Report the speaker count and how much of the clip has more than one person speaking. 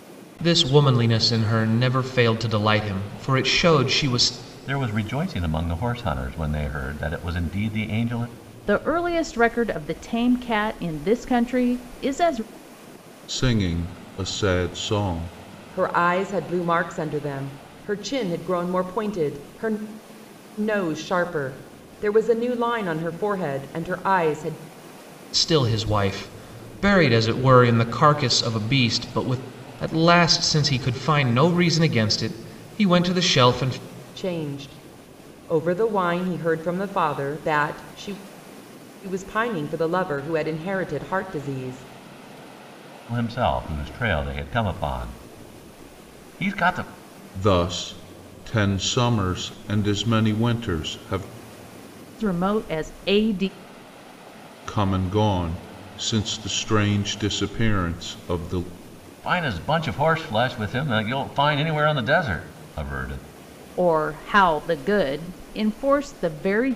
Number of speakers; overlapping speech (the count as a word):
five, no overlap